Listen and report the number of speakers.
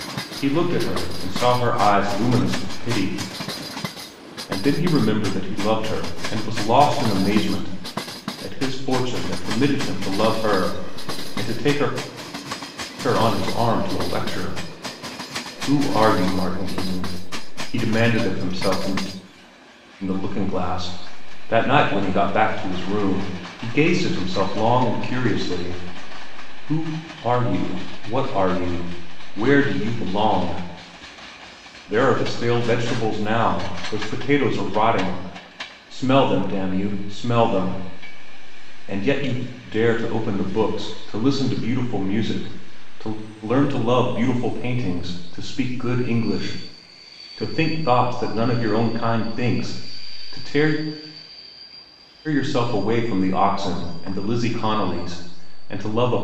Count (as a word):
one